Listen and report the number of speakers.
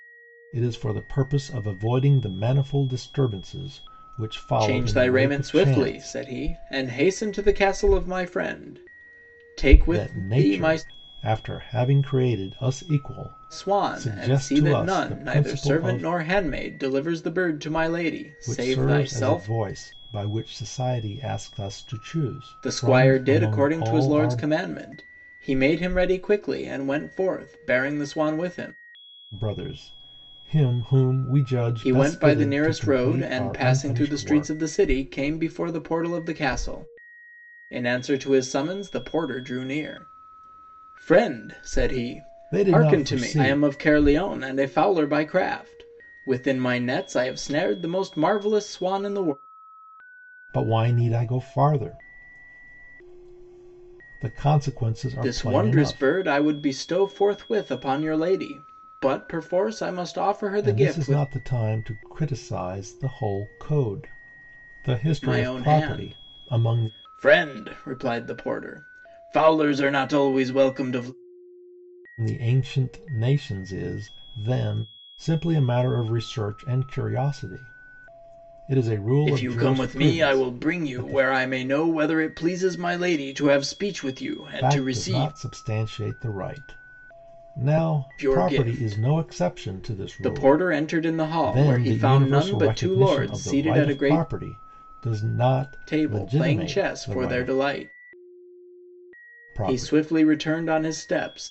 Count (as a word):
two